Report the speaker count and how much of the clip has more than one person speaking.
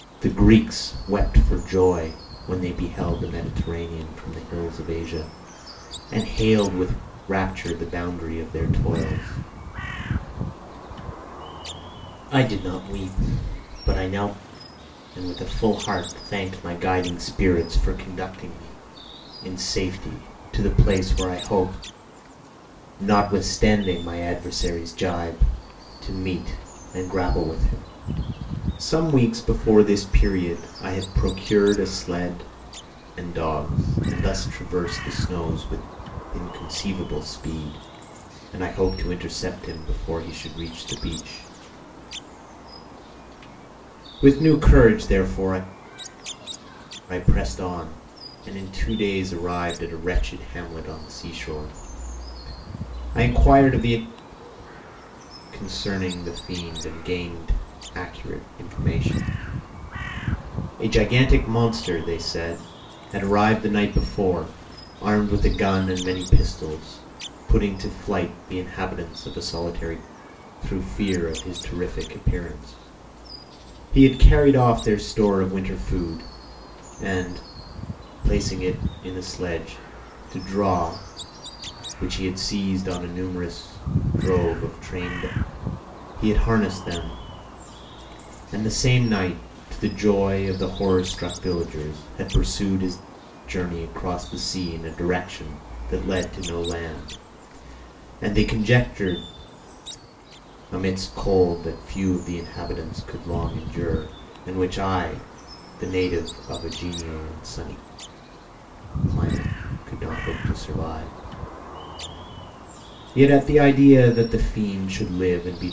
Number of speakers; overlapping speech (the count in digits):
1, no overlap